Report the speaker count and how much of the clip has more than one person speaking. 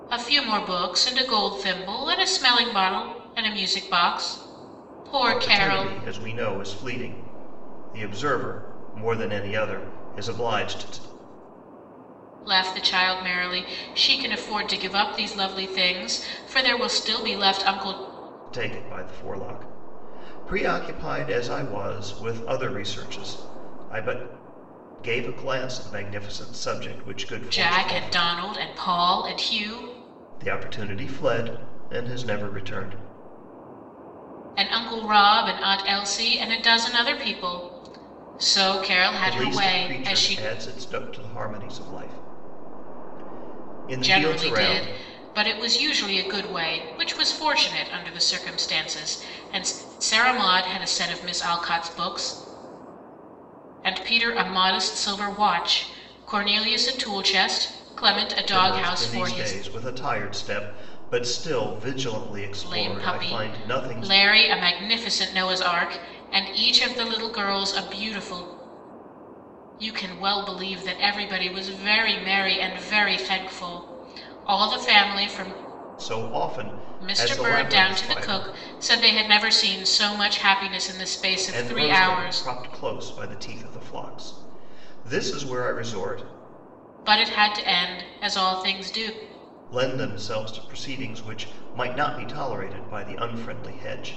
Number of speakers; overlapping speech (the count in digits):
2, about 10%